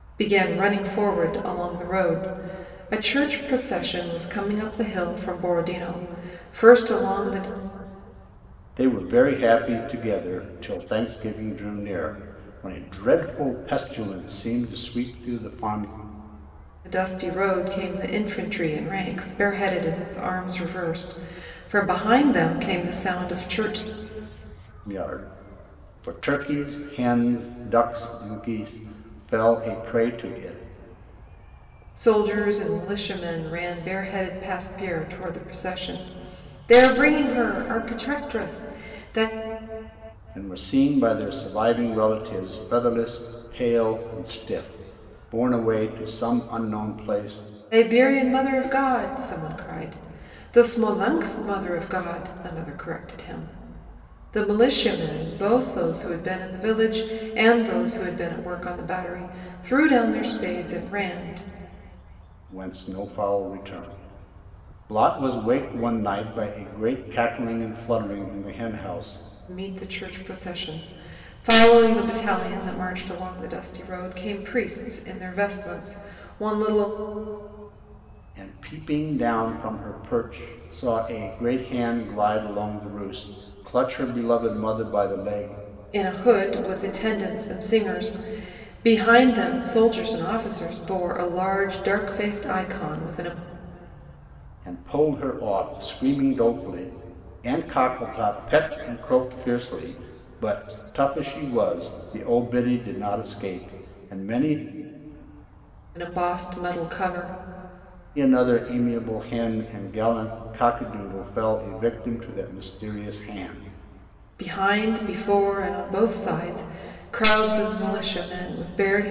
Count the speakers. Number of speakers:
2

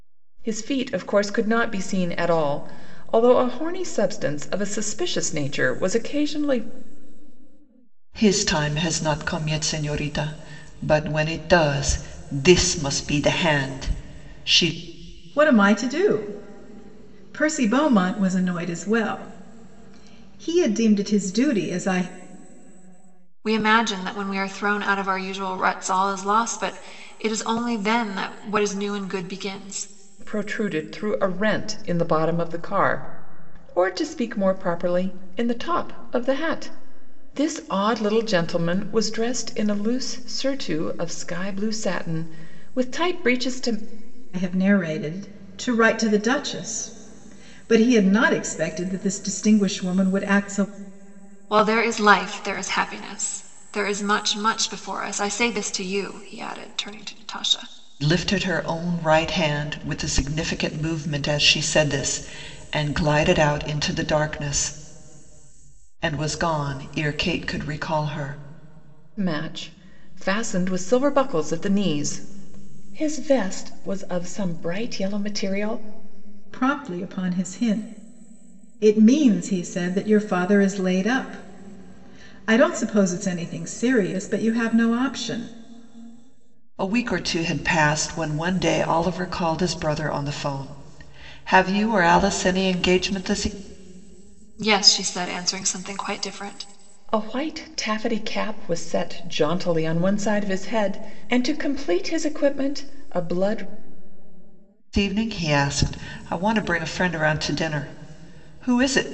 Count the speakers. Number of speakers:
4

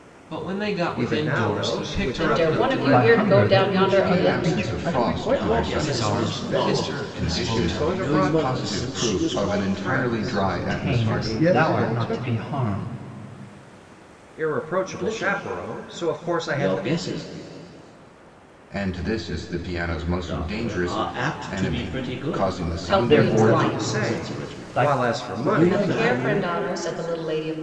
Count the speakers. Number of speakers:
7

